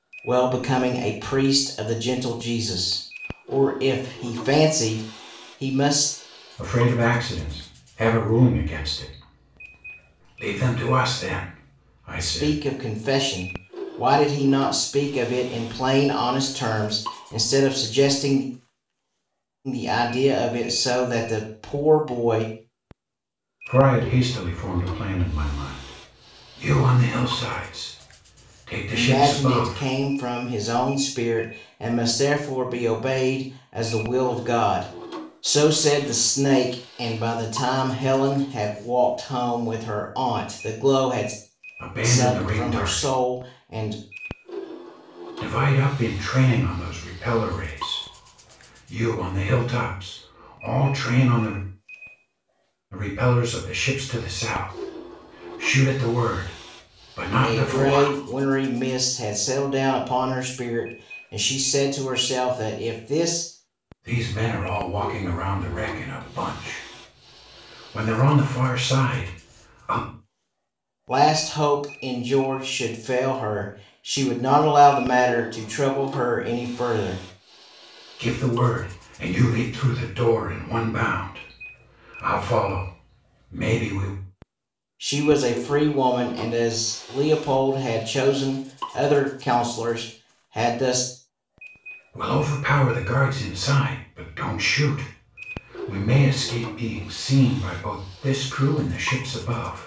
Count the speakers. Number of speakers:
2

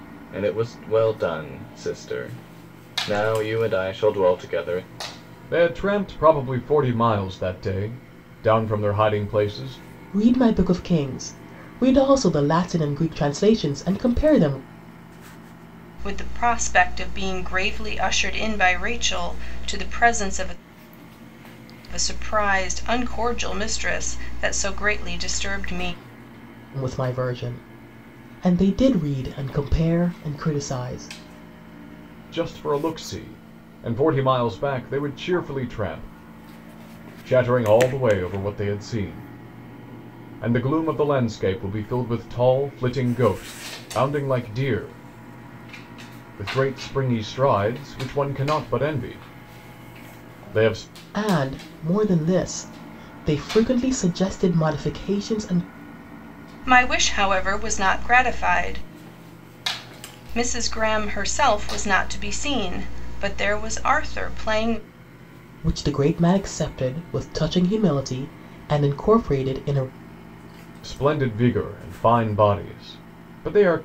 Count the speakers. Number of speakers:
4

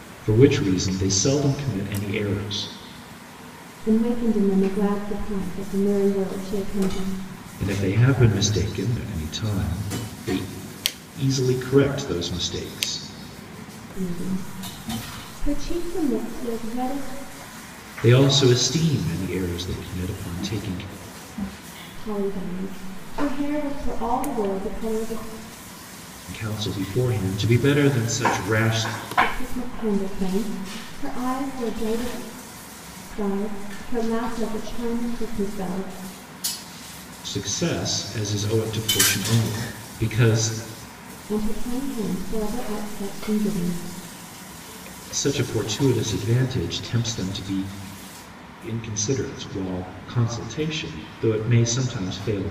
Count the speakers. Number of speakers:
2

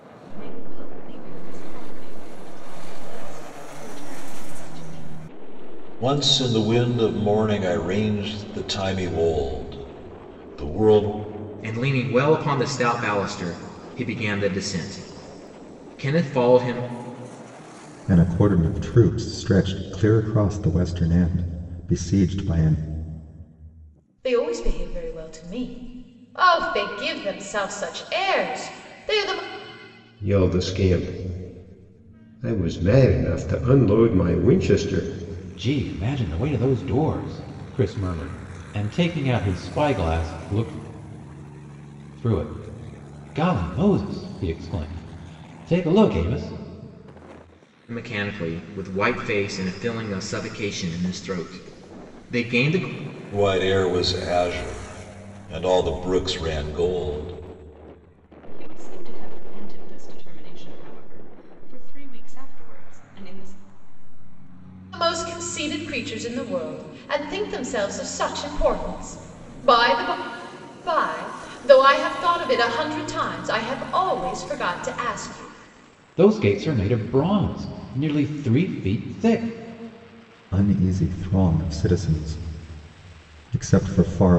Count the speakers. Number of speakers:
7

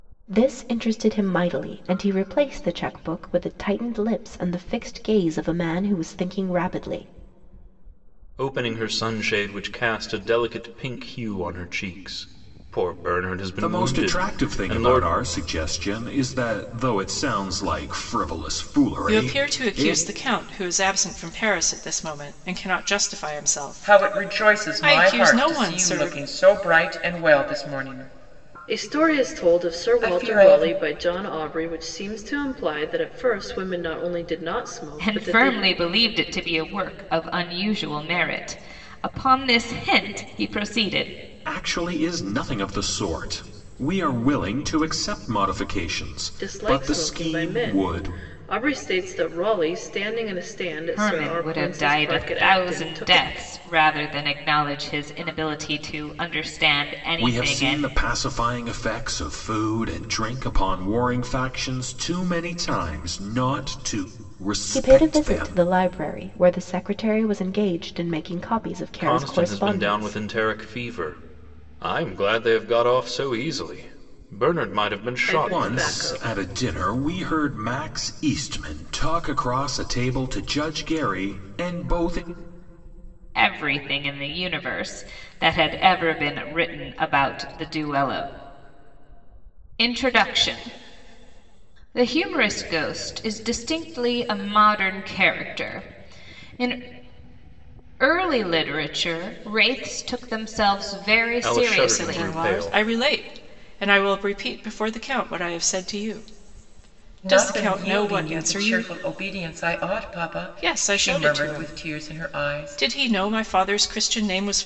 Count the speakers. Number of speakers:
7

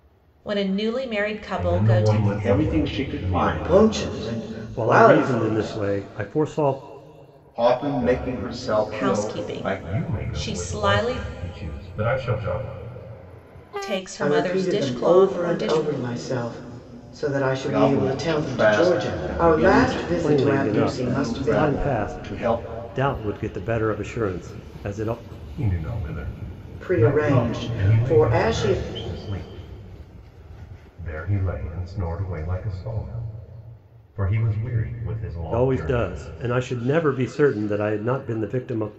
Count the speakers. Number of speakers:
5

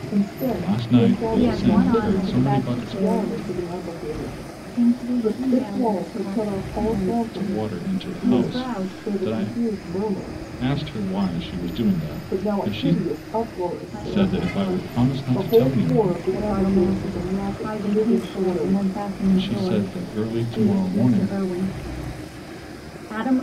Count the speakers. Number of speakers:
3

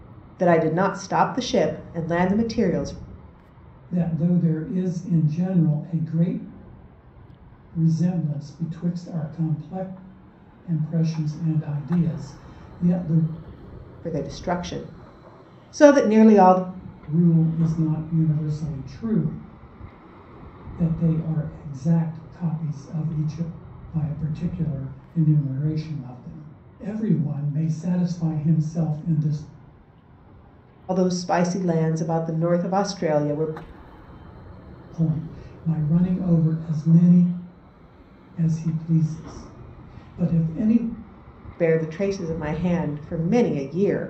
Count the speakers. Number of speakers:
2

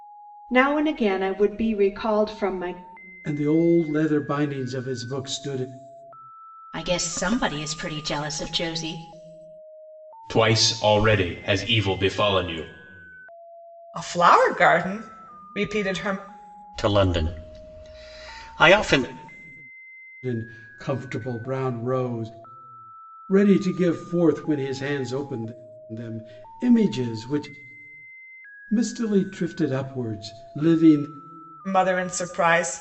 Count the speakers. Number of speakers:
6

